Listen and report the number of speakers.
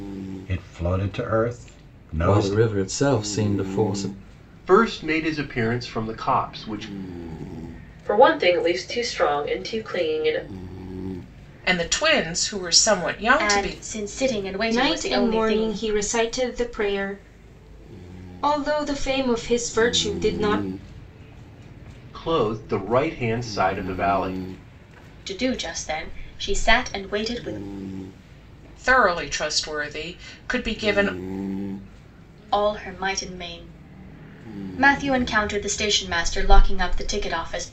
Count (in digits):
7